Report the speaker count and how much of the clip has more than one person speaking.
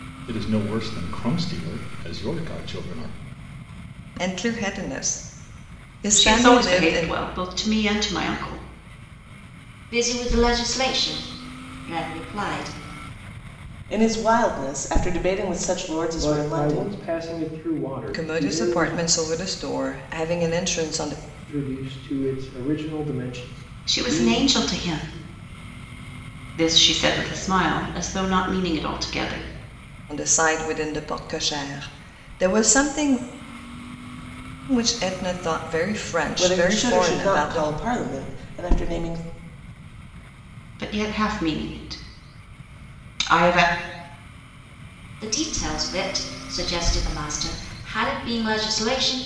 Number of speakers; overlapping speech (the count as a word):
six, about 10%